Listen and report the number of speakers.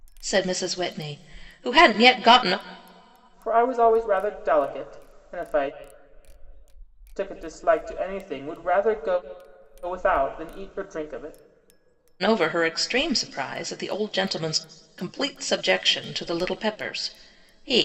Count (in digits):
2